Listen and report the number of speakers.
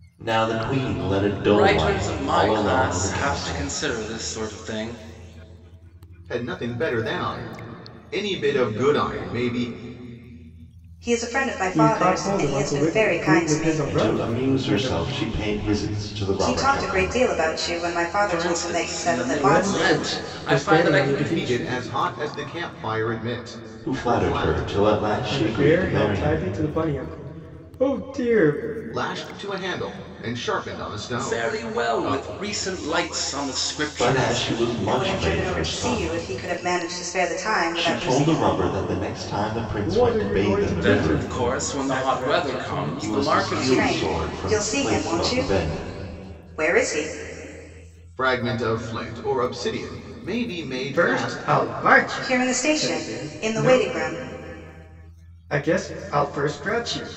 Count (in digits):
5